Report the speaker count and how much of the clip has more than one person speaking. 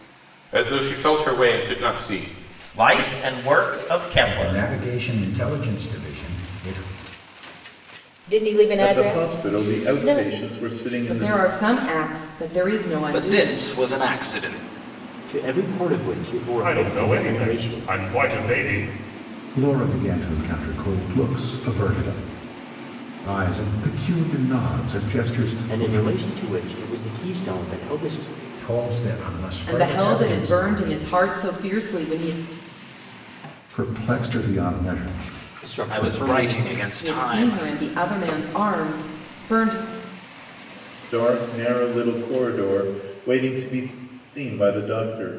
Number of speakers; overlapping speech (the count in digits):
10, about 20%